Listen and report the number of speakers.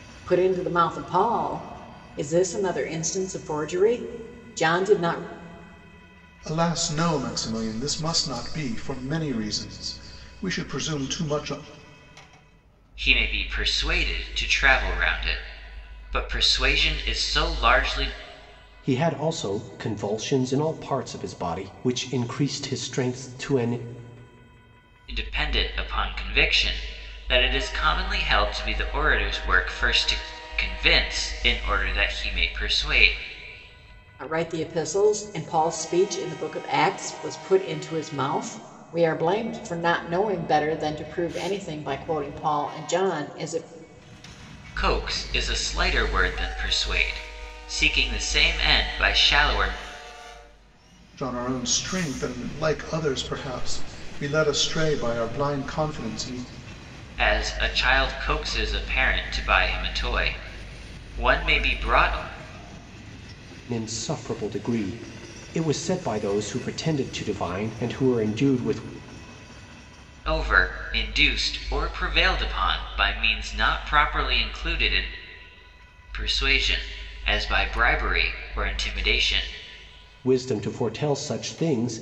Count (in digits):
4